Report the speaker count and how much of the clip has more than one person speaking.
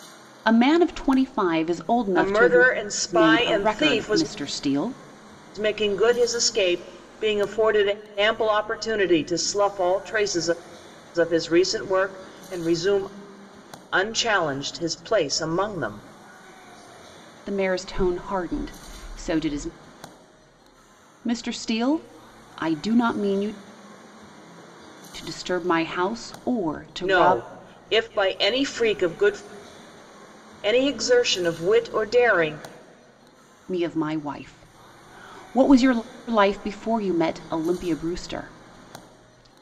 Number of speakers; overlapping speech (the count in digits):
2, about 6%